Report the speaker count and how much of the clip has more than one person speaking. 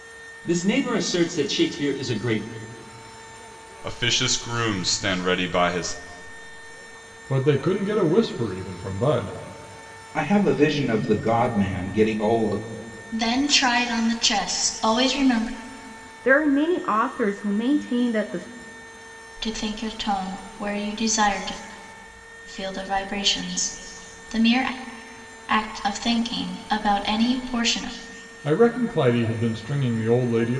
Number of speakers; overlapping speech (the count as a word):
six, no overlap